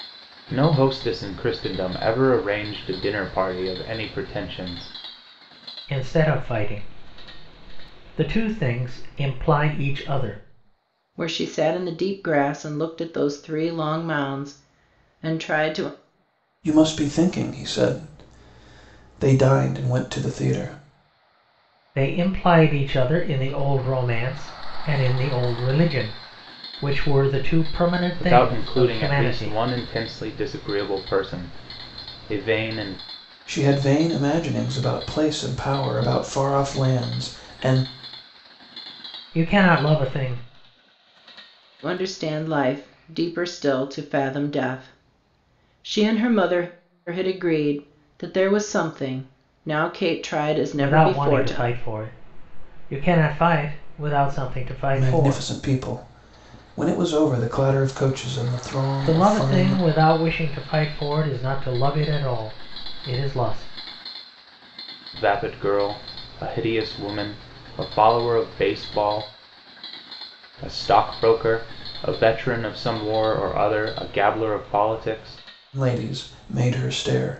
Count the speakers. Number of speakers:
4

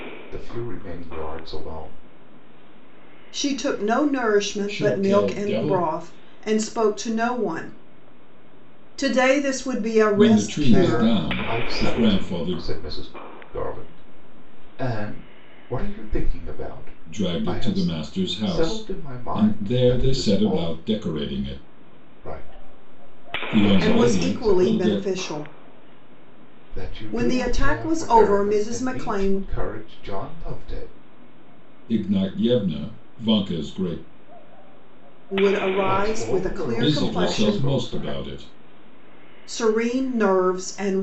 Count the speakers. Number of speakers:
3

